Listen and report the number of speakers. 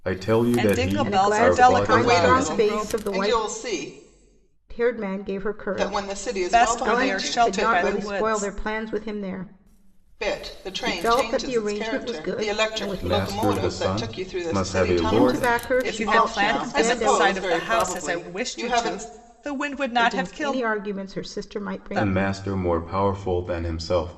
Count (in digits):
4